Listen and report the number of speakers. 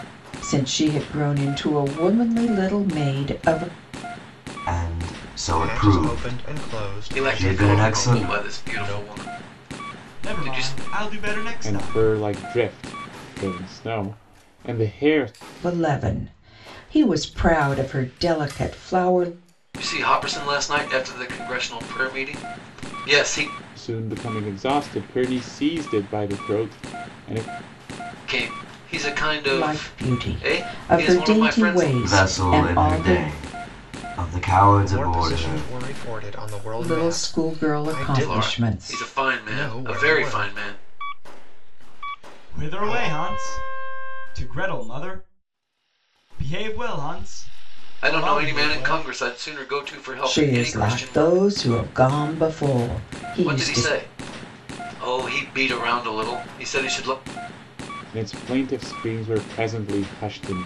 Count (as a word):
six